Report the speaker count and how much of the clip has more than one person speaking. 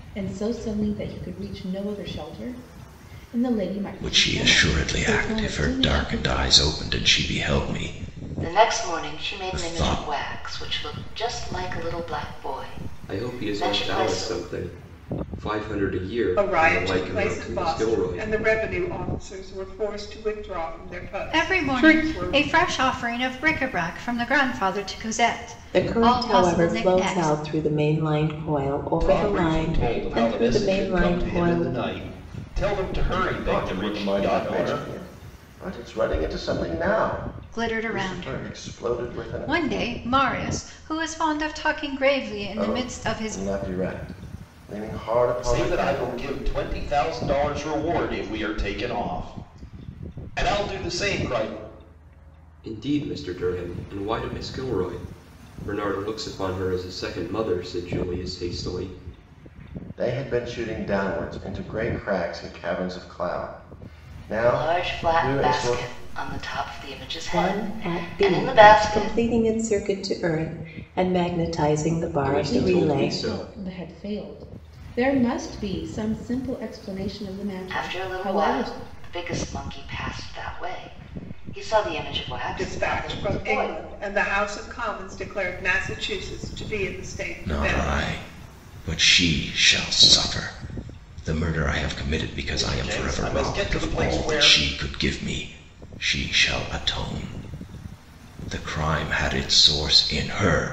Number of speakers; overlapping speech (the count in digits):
9, about 28%